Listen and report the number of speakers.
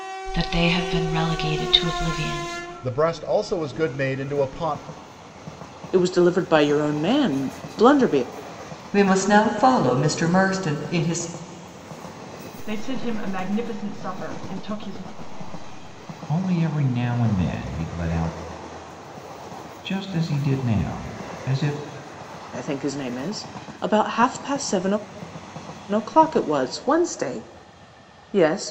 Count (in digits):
6